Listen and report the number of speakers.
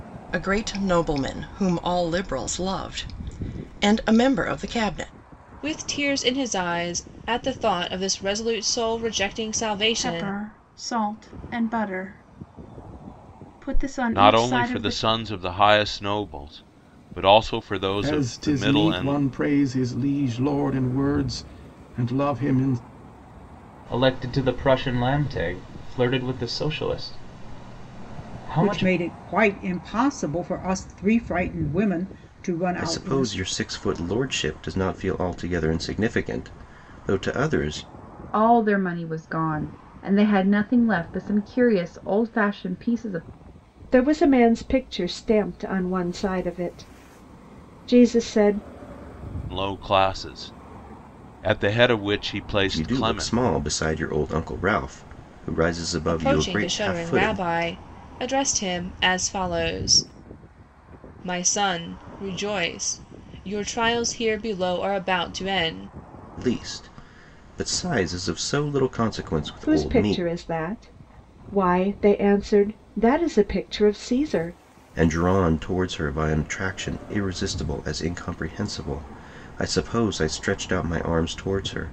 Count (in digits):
10